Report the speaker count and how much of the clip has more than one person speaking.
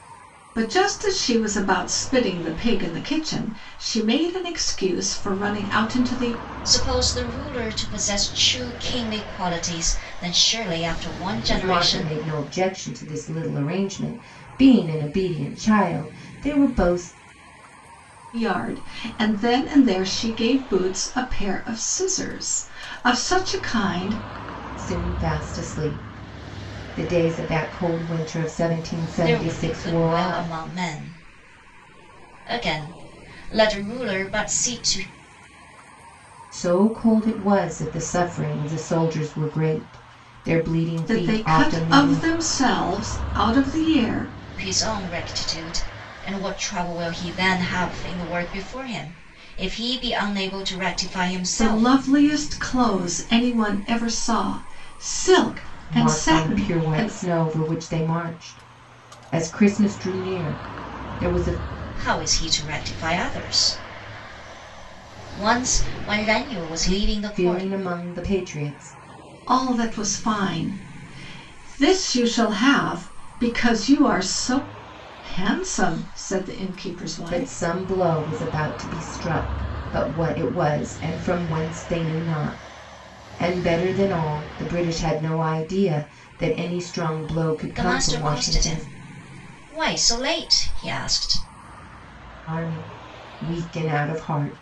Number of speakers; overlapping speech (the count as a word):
three, about 8%